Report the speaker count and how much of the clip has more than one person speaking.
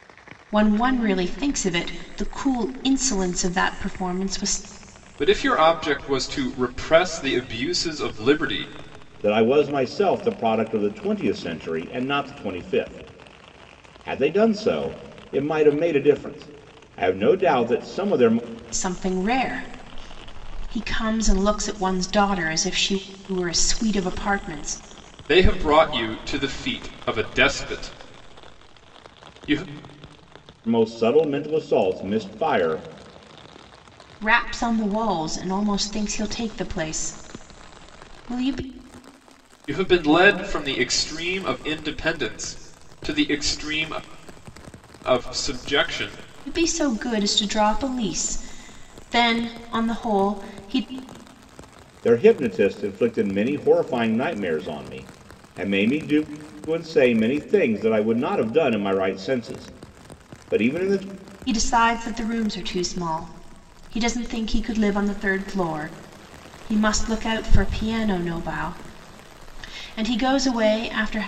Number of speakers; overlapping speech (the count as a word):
three, no overlap